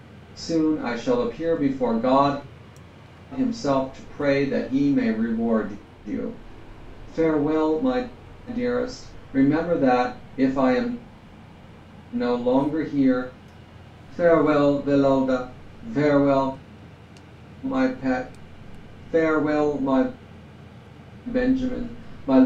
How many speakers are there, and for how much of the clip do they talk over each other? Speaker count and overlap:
1, no overlap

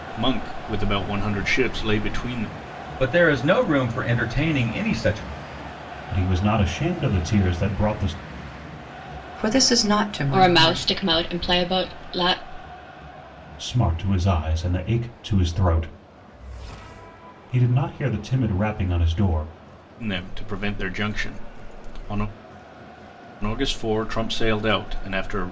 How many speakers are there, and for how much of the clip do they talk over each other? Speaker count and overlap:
5, about 3%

